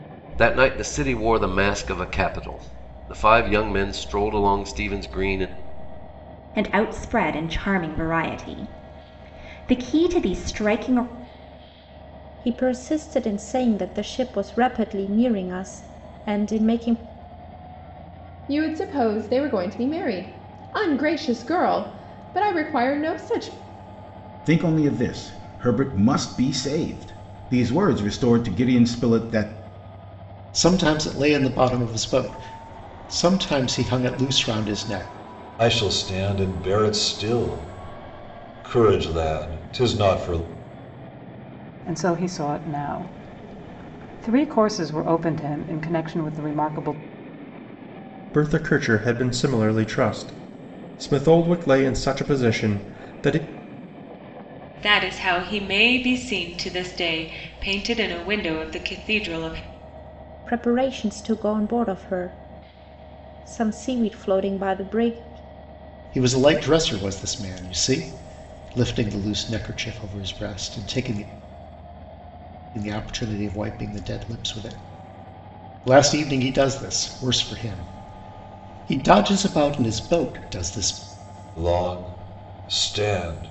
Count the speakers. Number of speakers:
10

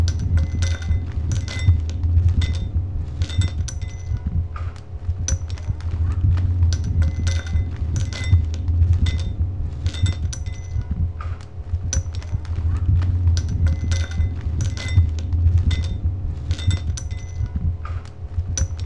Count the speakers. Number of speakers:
0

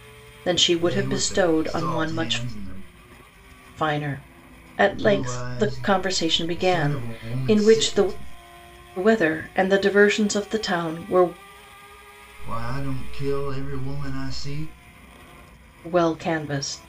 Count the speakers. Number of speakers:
2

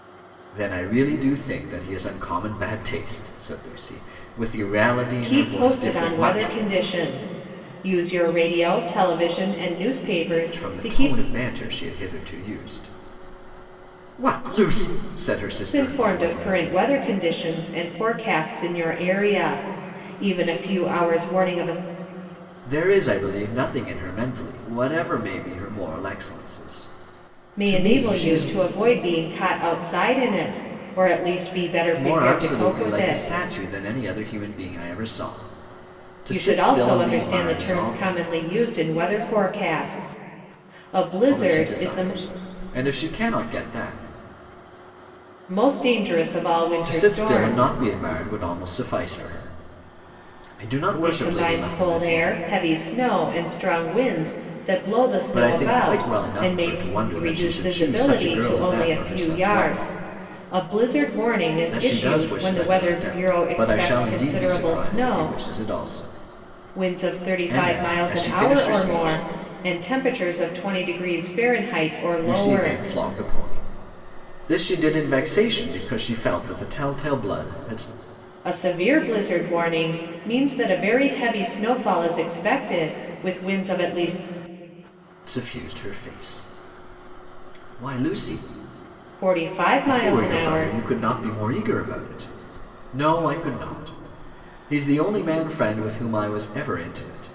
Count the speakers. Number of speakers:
2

